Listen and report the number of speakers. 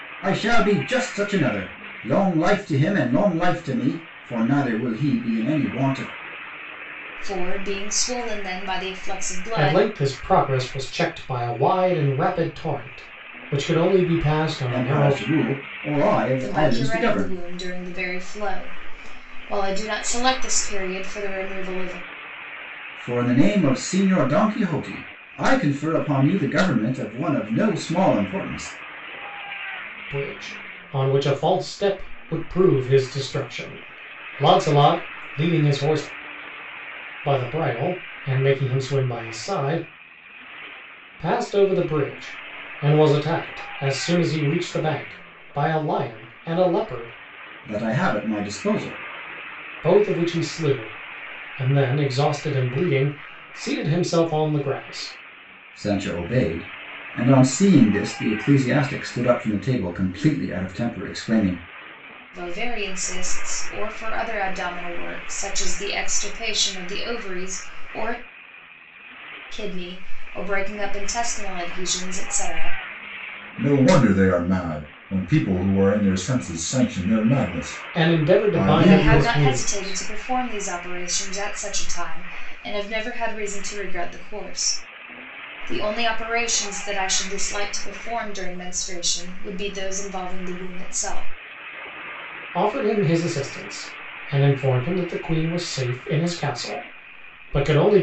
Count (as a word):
three